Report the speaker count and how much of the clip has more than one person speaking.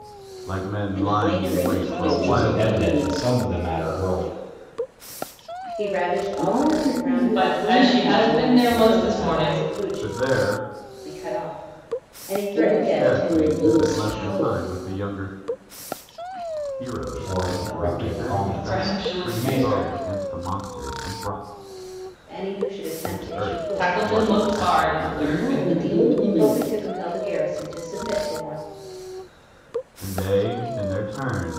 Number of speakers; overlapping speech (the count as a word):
six, about 47%